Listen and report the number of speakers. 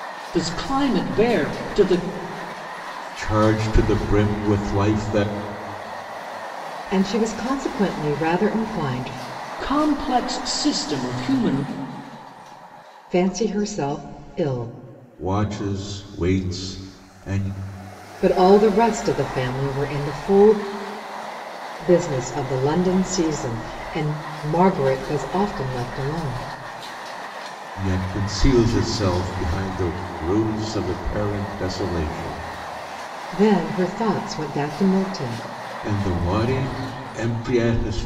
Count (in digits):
3